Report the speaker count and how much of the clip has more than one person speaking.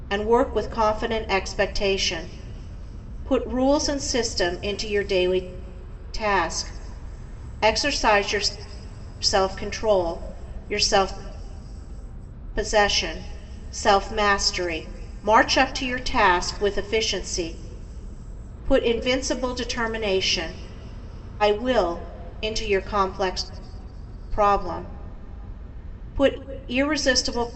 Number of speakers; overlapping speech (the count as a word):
one, no overlap